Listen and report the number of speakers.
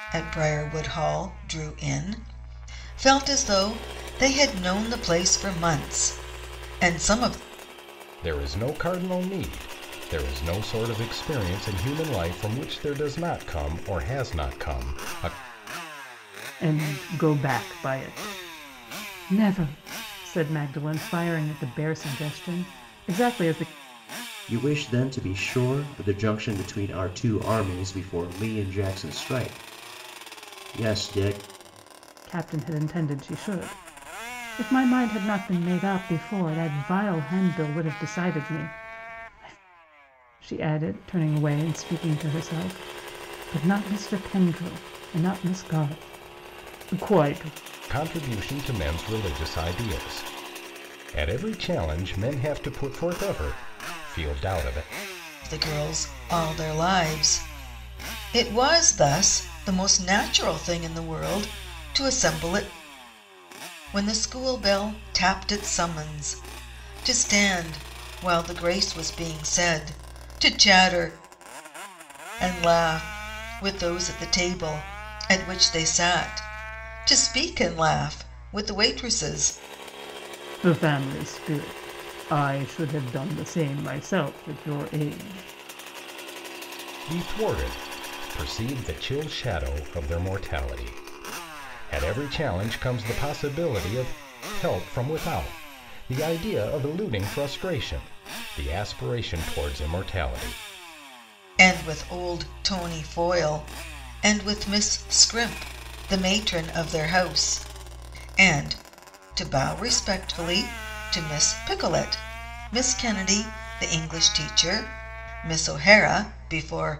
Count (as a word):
four